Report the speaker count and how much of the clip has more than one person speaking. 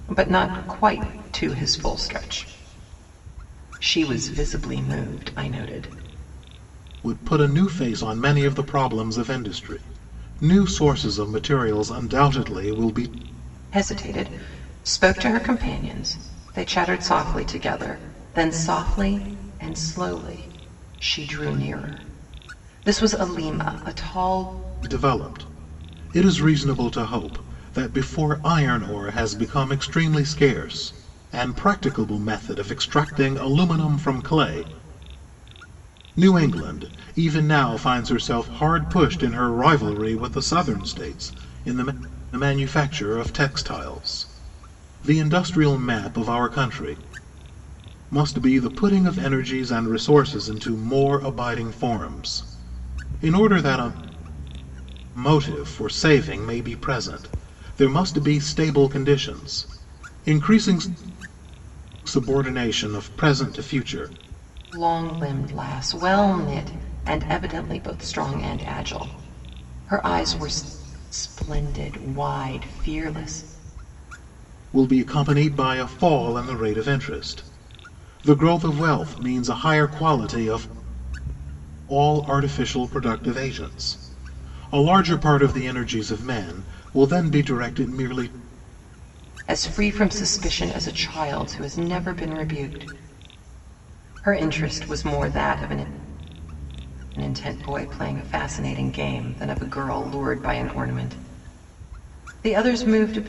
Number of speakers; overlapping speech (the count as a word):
two, no overlap